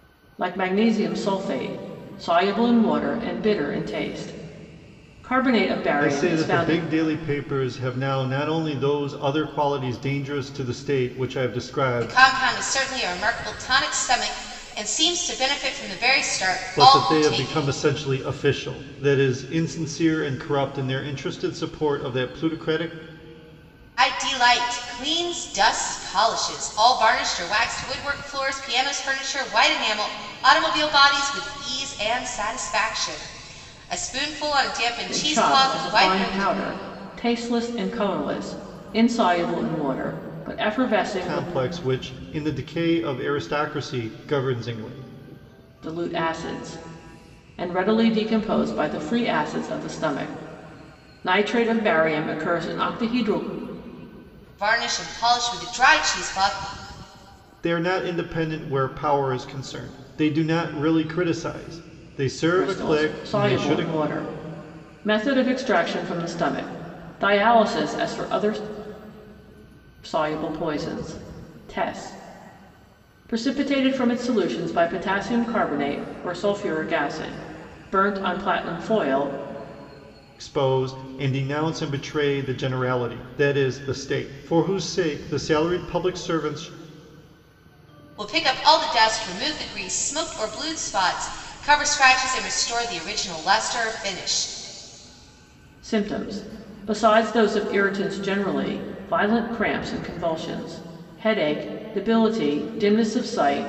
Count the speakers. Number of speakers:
three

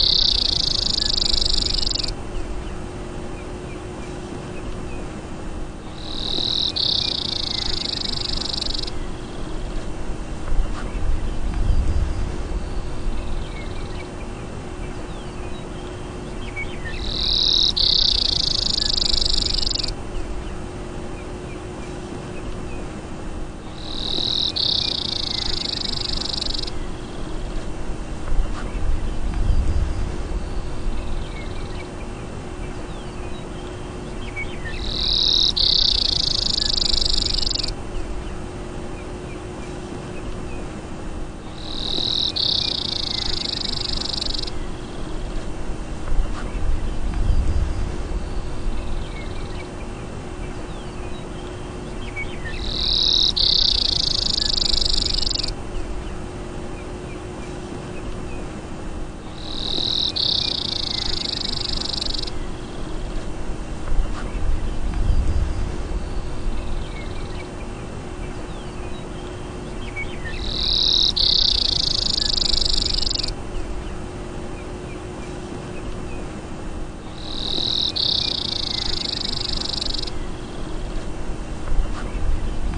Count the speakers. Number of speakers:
zero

